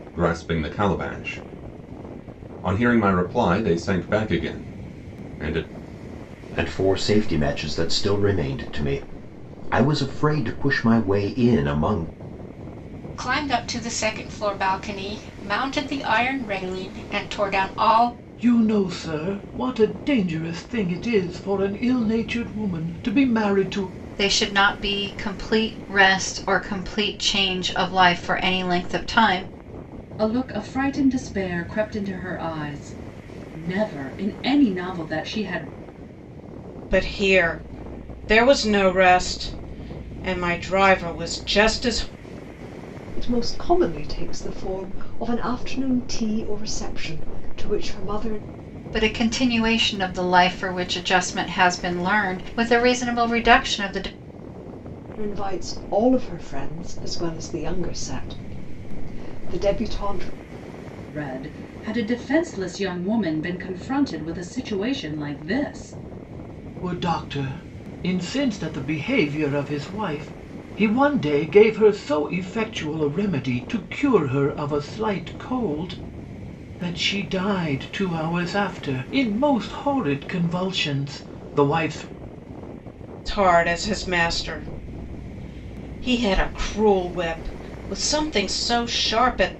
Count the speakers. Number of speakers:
8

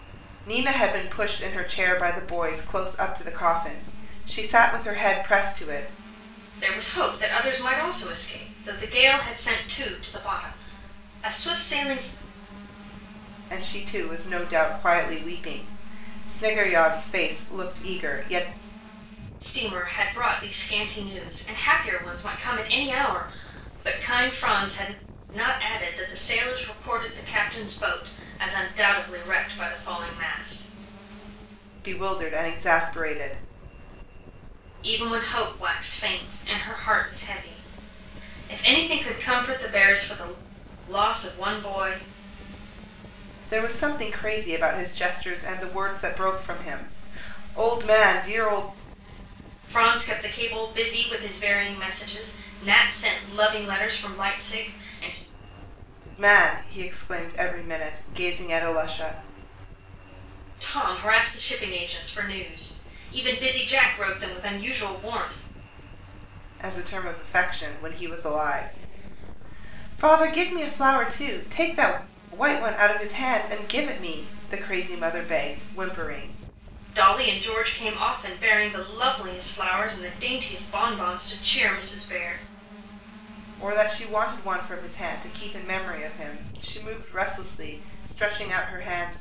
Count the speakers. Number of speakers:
2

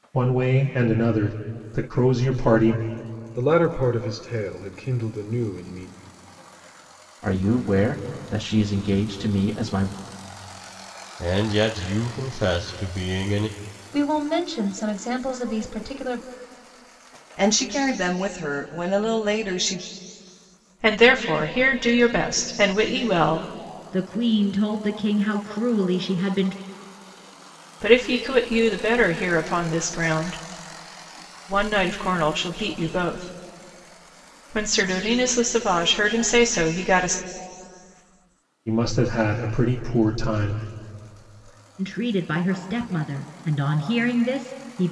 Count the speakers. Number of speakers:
8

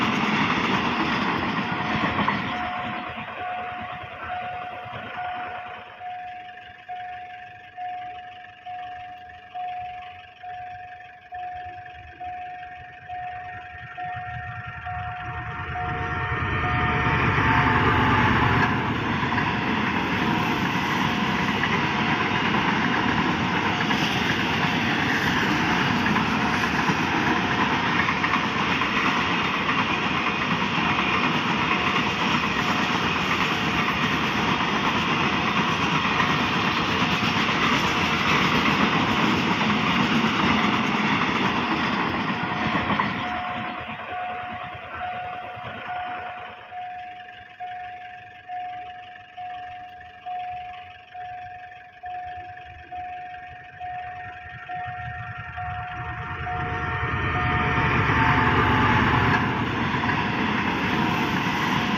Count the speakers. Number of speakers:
0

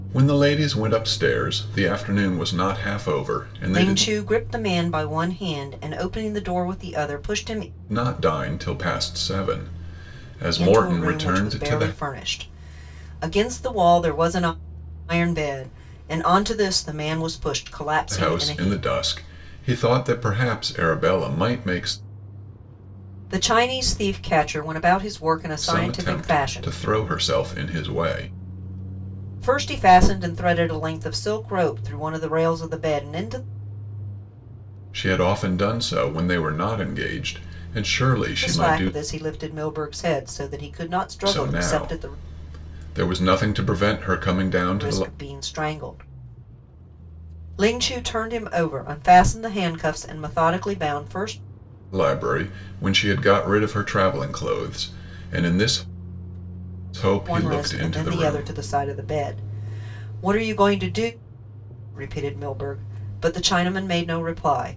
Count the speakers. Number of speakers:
2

